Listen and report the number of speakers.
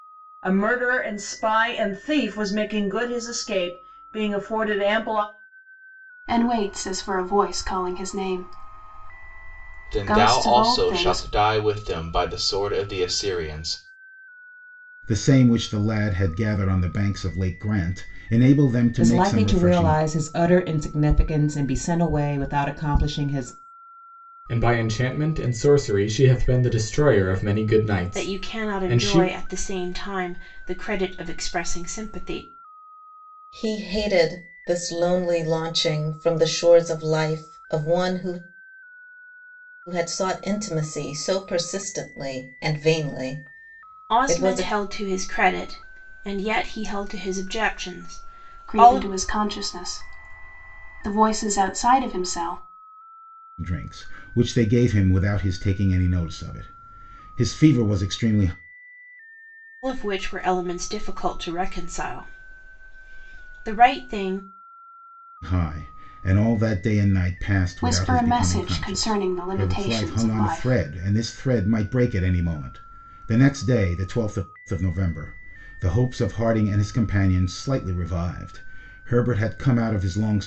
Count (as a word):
eight